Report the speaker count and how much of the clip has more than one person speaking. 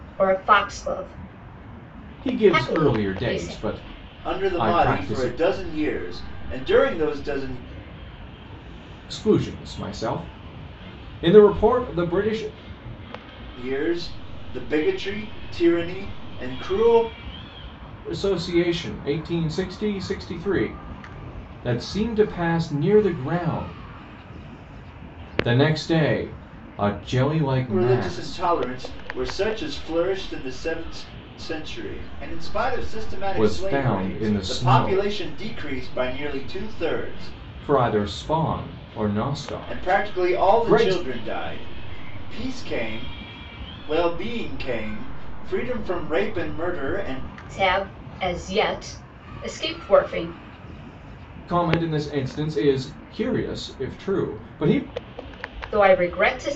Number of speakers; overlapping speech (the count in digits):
3, about 11%